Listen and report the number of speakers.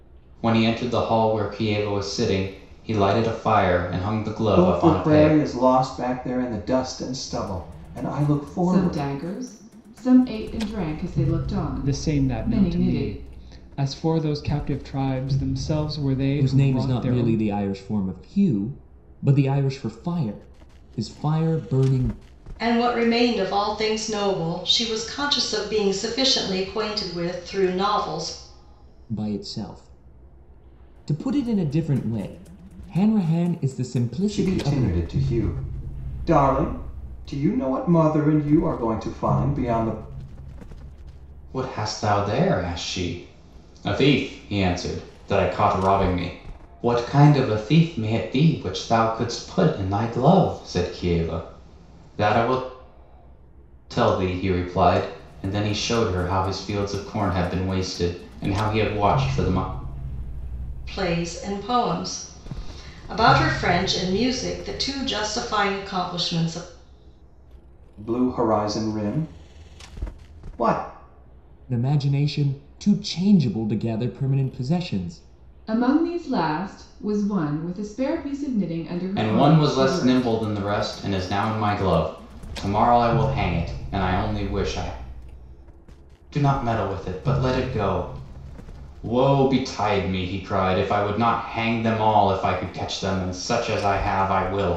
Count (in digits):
6